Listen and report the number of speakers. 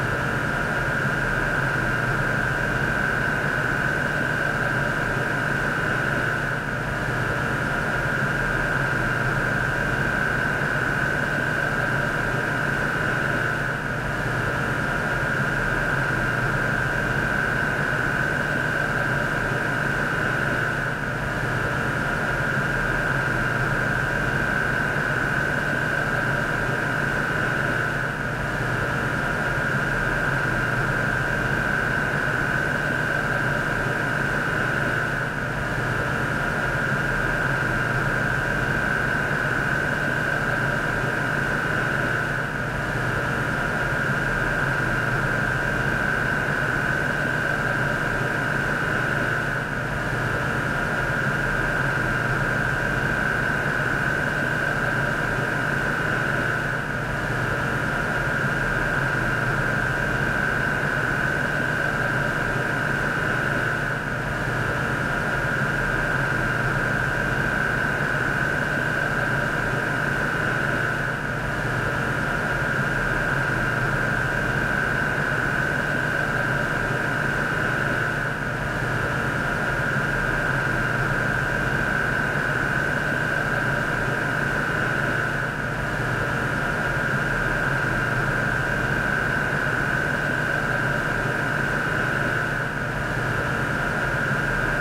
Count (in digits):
0